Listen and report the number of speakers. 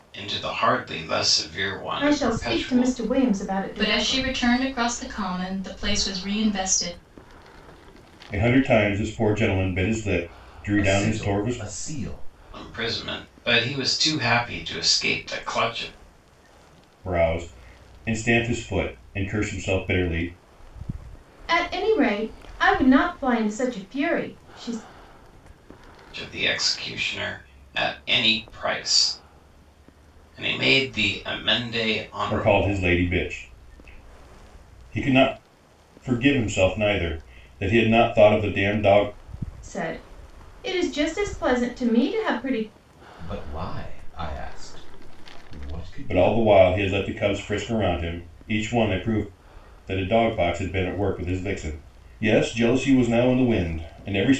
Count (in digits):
5